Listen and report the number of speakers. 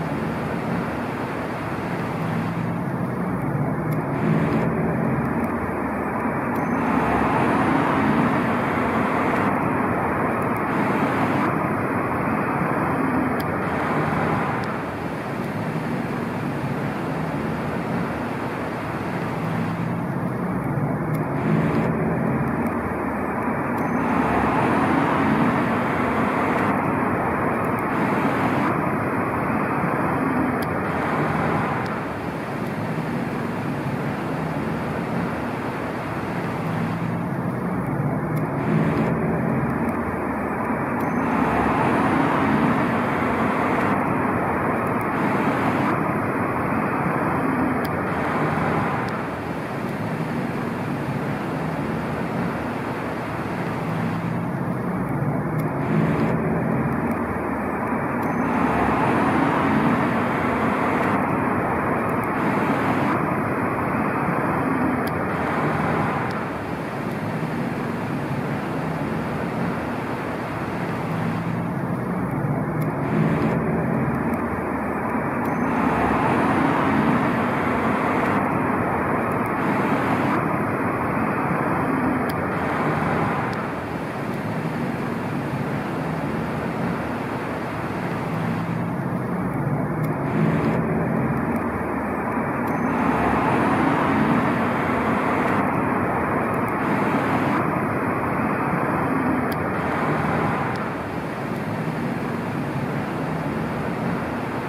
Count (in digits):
0